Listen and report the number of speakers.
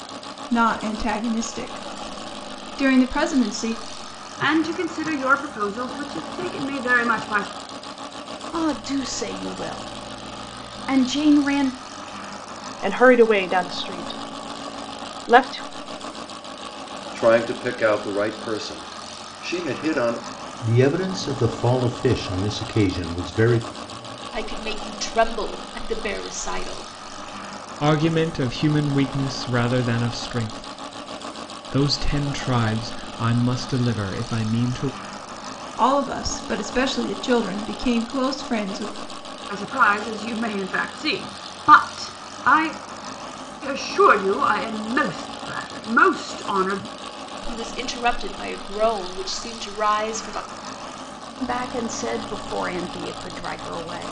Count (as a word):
eight